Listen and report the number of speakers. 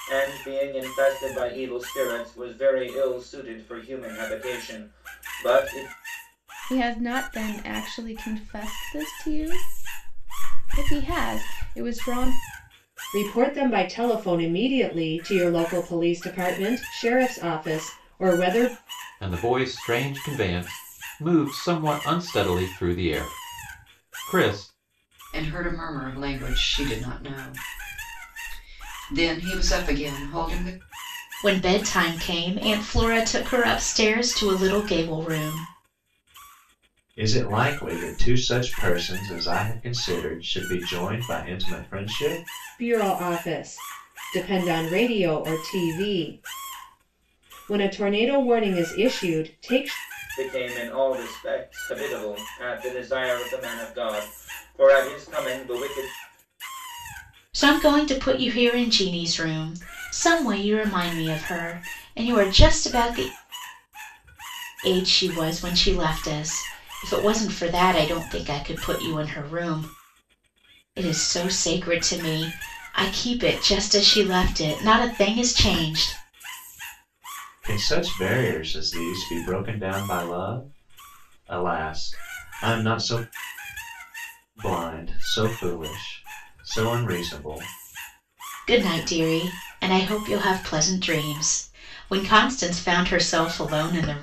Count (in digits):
7